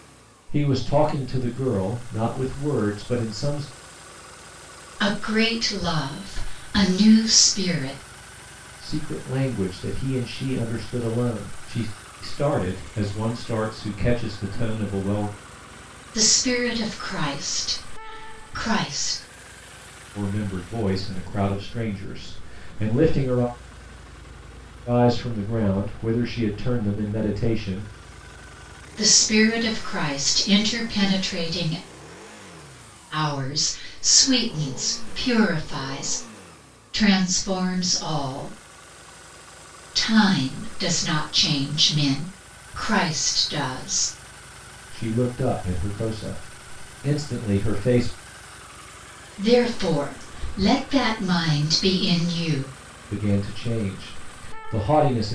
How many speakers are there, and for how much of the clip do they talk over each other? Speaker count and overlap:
2, no overlap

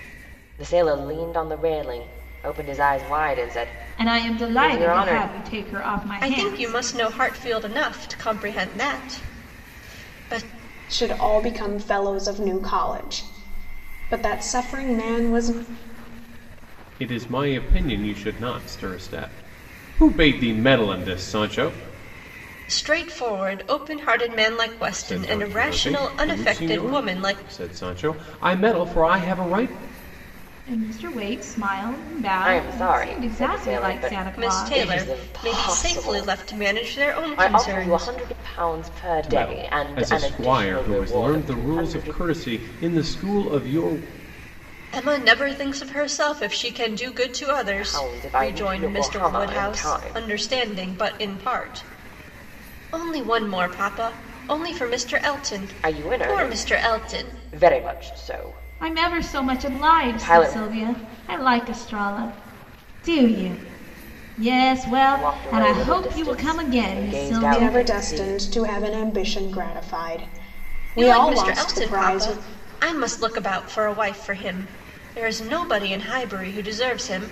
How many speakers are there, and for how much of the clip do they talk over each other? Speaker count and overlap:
5, about 29%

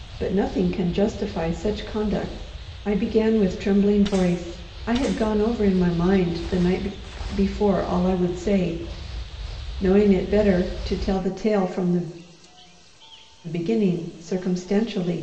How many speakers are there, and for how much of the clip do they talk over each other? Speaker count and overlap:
1, no overlap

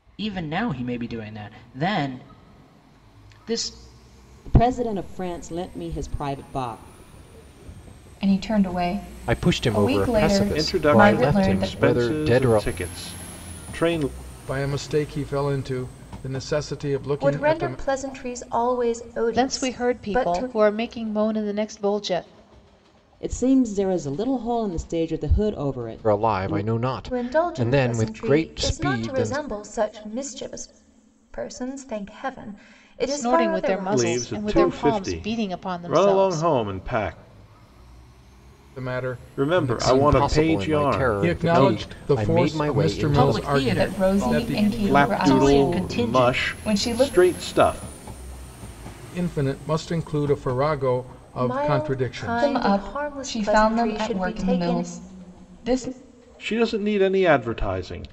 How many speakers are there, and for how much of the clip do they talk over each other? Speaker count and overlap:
8, about 39%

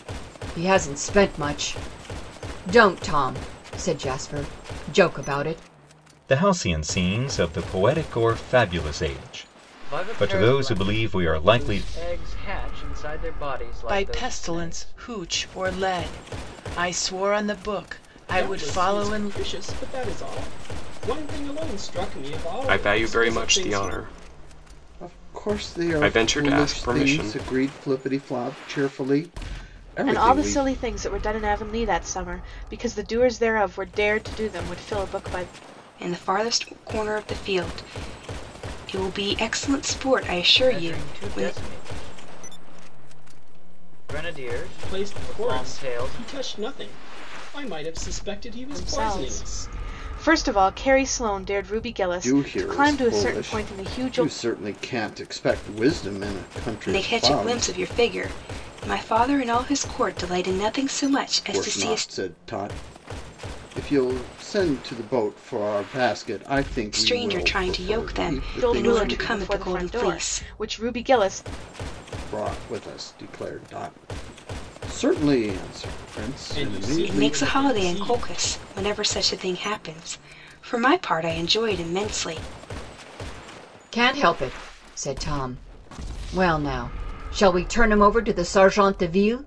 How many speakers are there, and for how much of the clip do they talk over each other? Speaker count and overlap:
9, about 24%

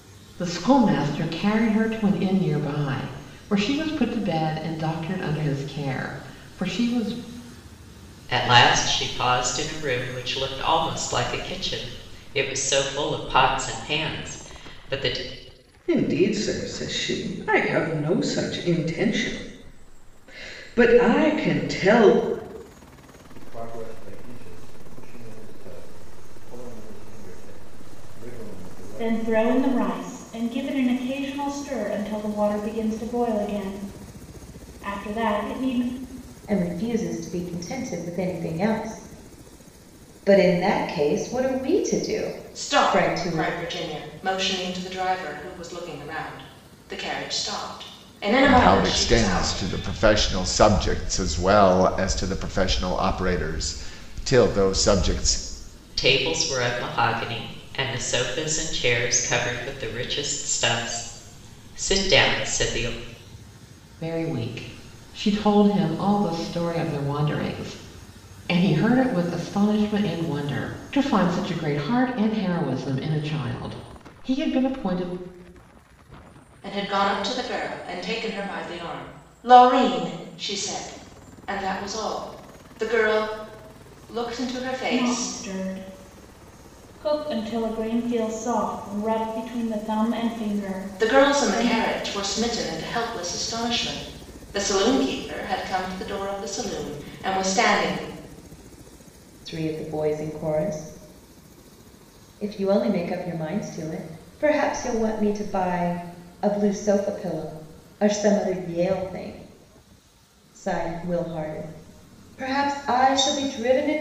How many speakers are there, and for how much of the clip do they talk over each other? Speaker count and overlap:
8, about 4%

